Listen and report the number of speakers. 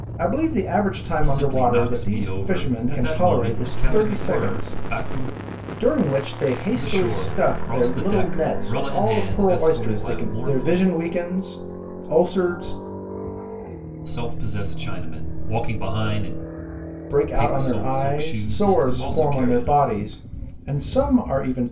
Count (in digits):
2